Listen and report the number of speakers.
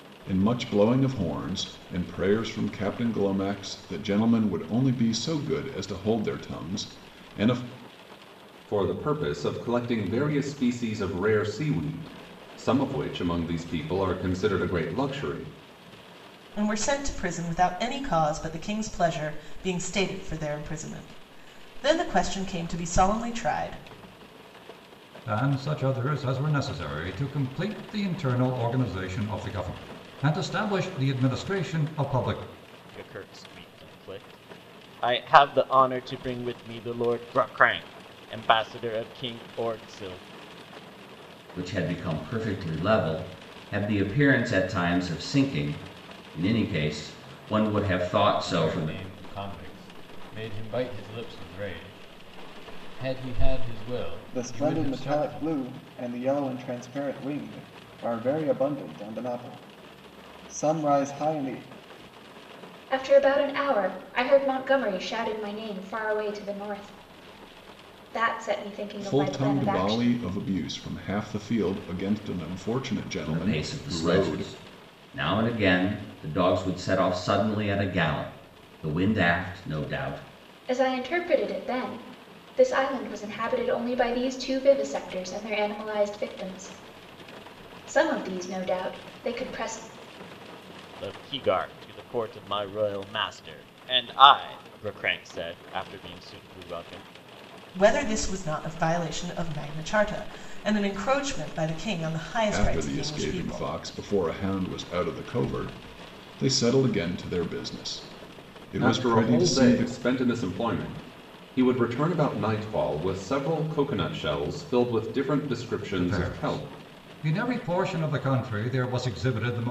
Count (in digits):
9